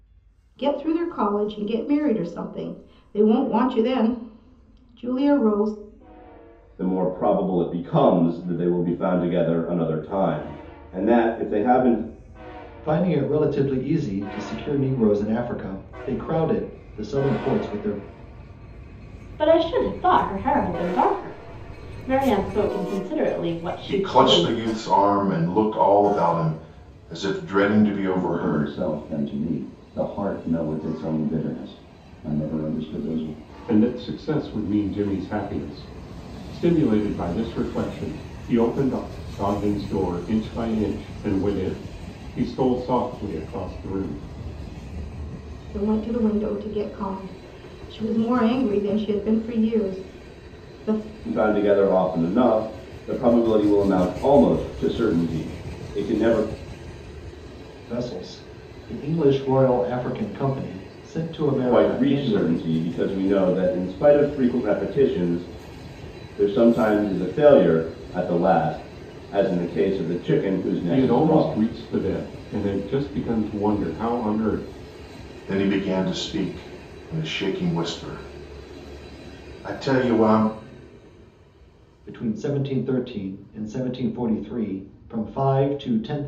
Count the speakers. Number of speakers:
seven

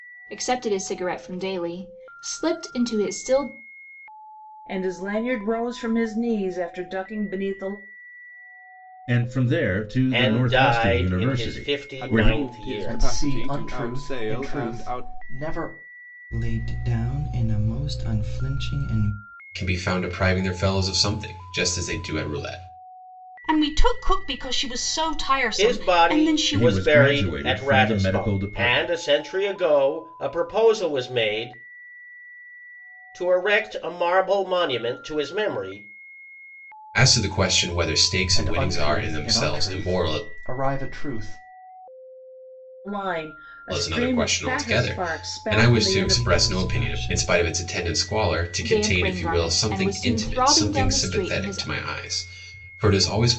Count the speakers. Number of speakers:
nine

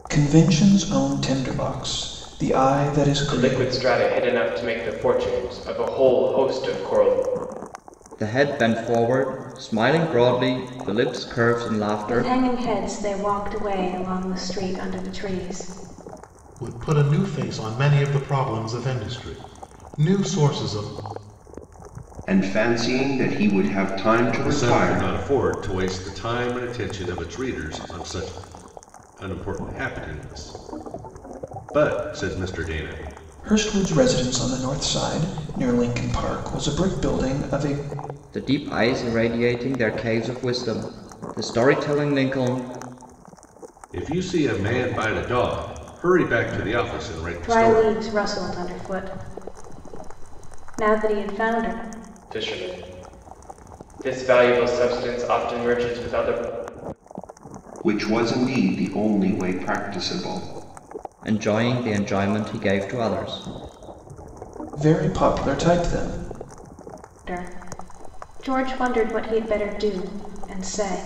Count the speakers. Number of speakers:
seven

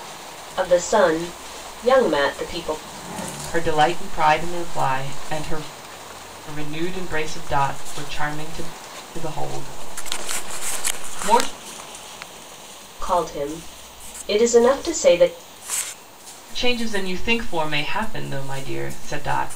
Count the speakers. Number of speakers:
two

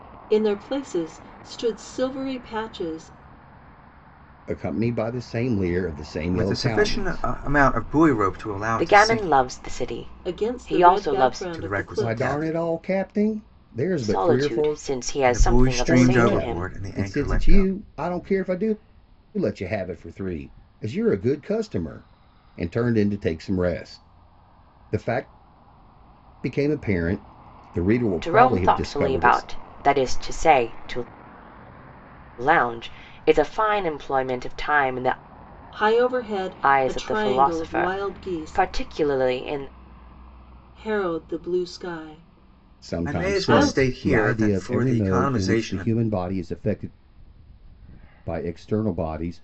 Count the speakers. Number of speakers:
four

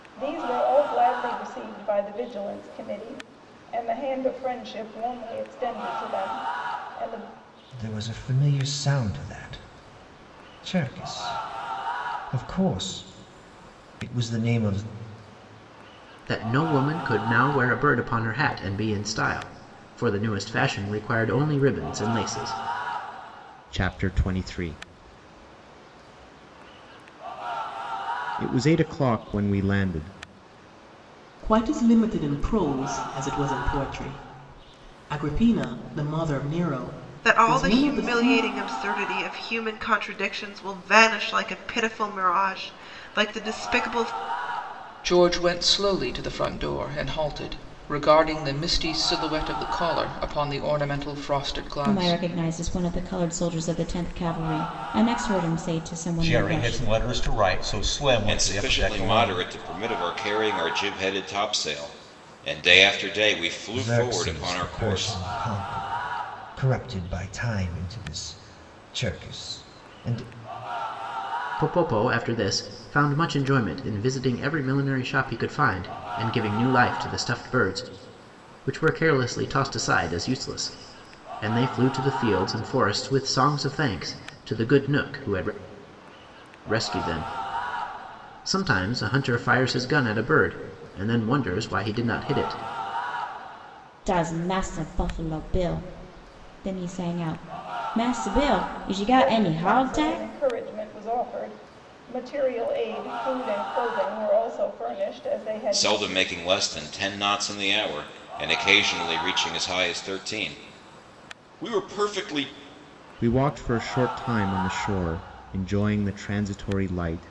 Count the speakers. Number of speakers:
ten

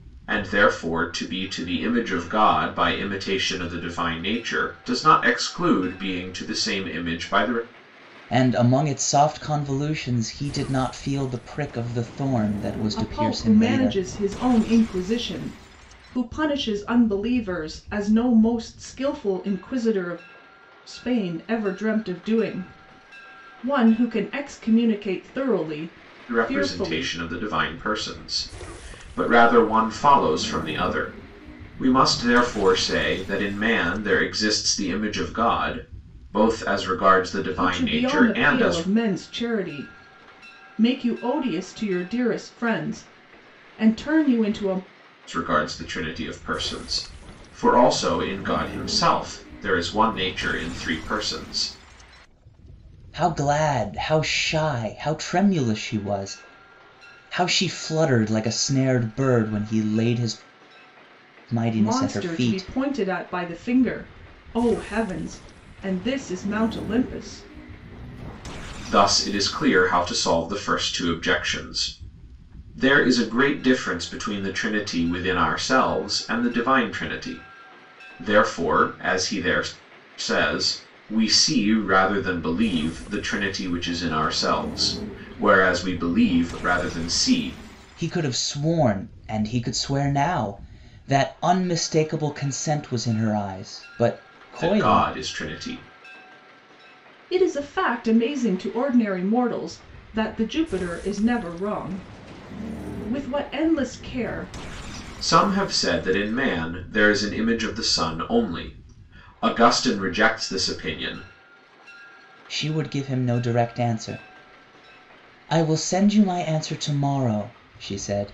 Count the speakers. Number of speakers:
three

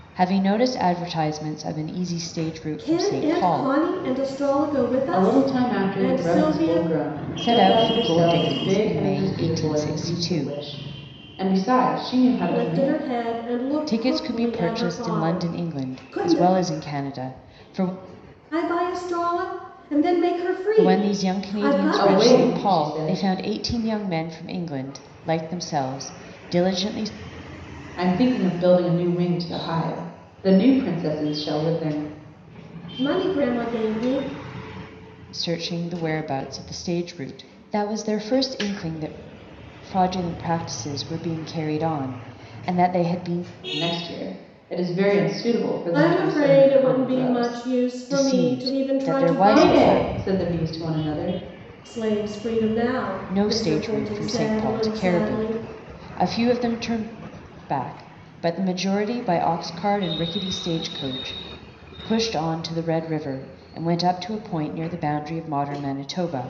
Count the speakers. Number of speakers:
three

